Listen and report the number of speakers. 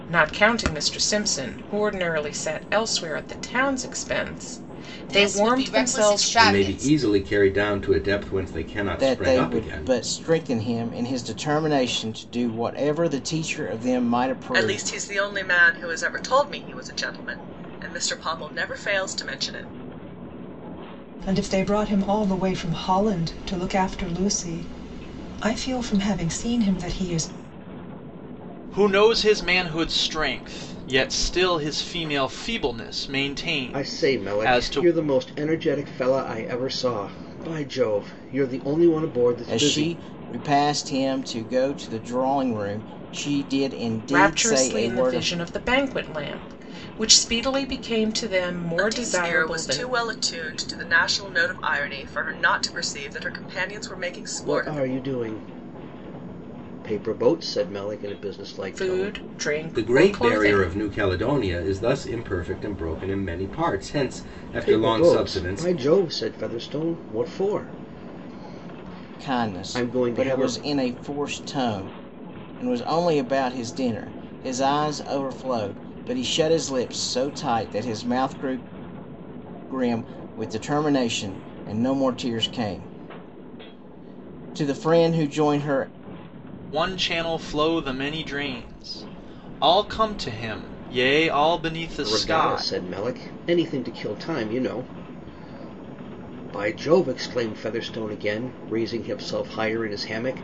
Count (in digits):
8